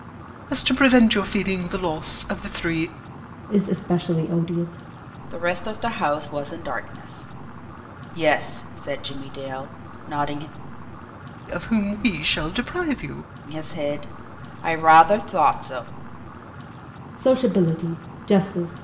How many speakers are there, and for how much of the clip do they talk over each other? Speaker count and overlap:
three, no overlap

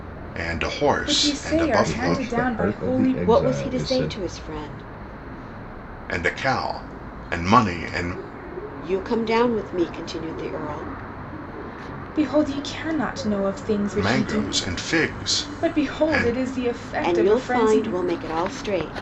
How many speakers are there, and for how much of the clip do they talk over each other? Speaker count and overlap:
four, about 29%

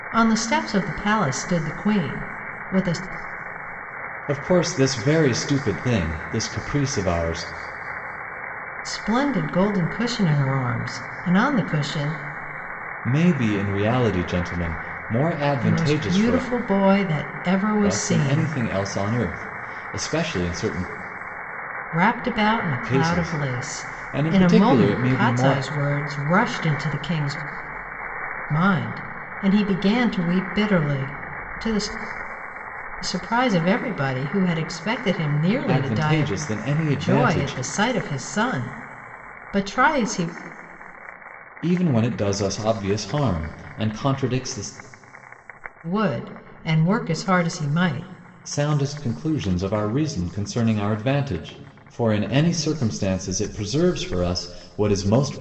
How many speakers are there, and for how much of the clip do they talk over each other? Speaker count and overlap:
two, about 10%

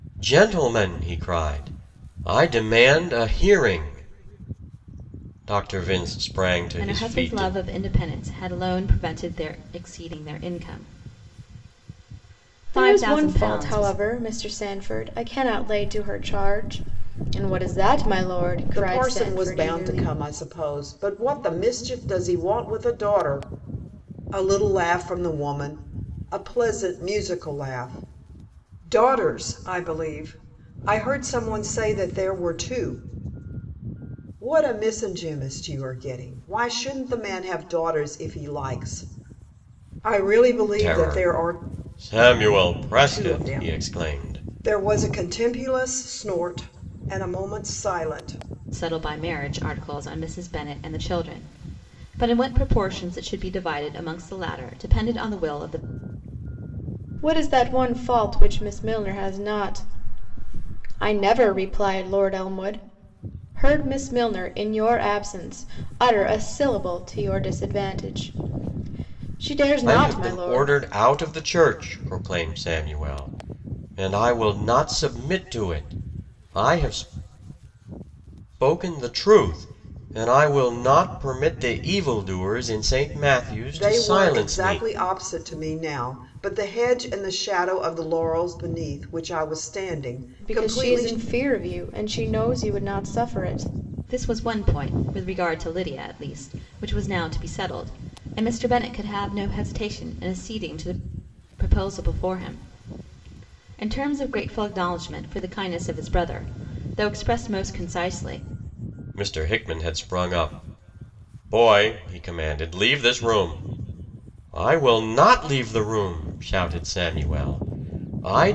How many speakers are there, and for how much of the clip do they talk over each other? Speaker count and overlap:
four, about 7%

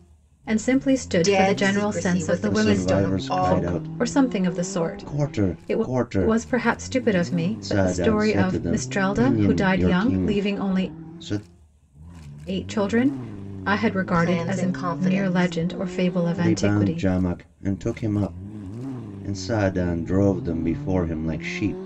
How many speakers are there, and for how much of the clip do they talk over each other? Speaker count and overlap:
three, about 44%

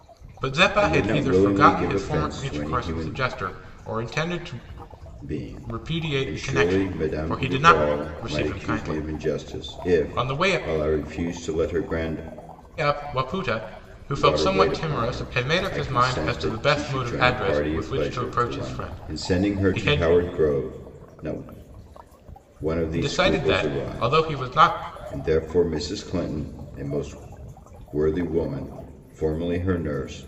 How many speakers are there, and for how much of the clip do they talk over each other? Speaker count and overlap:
two, about 47%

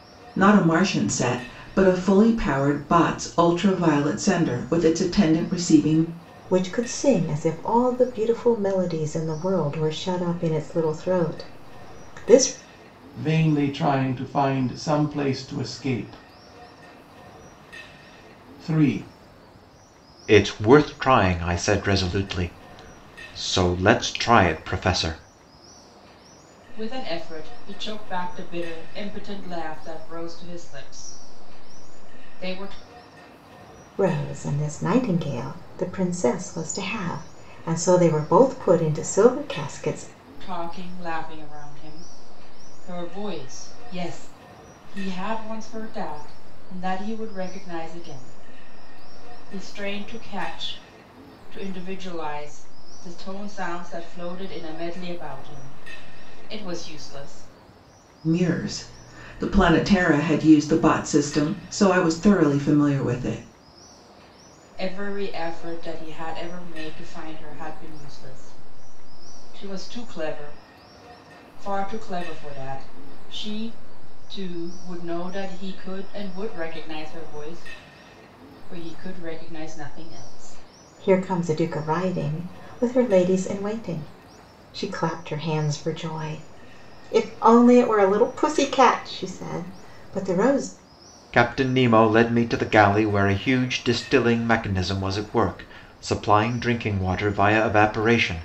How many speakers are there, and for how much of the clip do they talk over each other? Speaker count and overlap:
five, no overlap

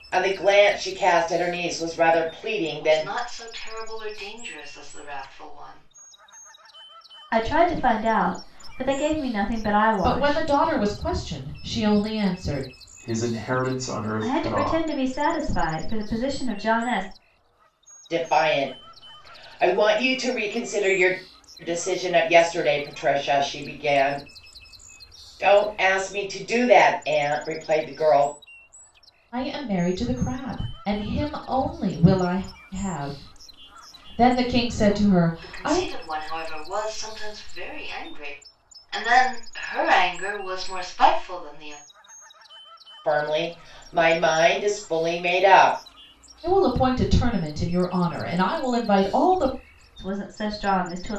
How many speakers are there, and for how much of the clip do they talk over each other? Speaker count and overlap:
five, about 4%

